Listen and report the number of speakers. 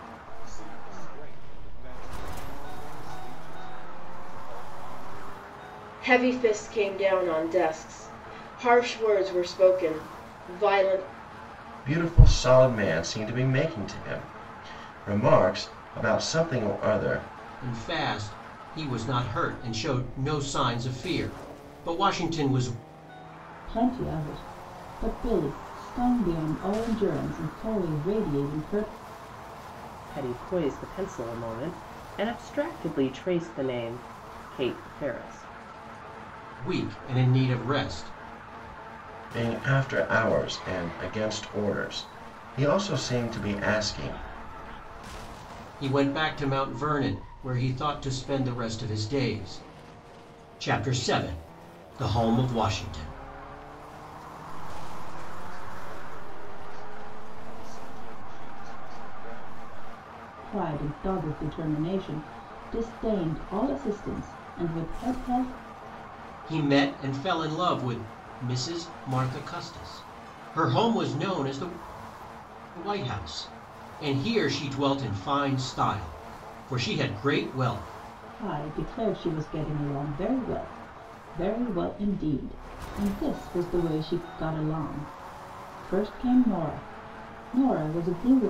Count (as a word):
six